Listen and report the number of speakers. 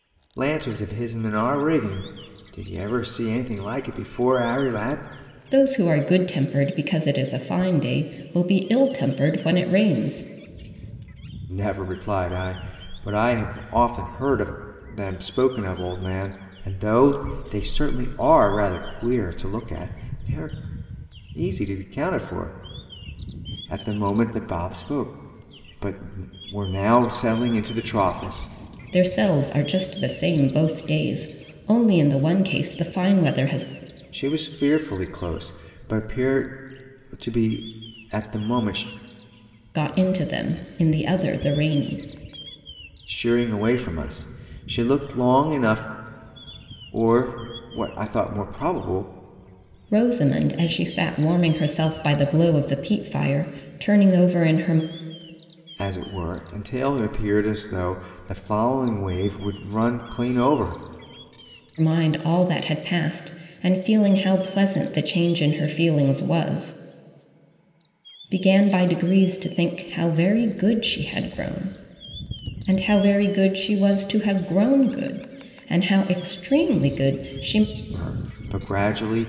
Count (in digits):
2